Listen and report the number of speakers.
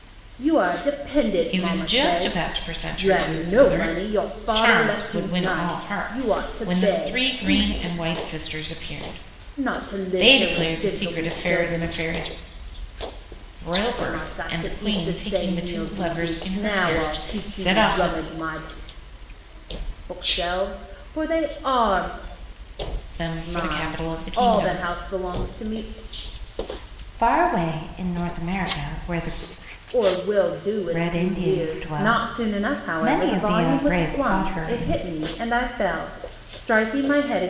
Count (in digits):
2